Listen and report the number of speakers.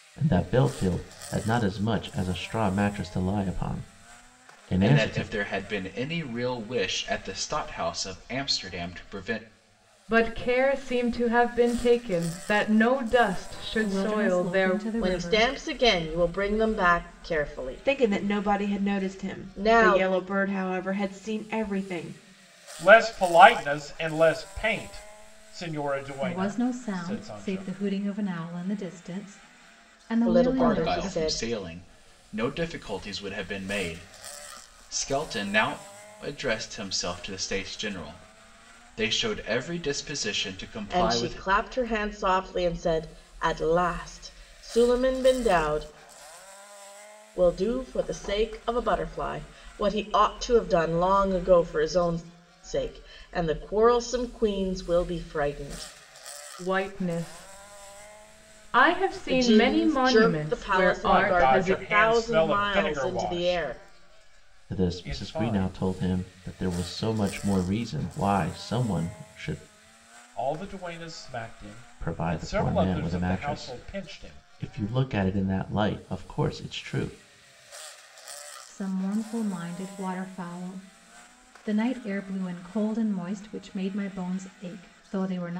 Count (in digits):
7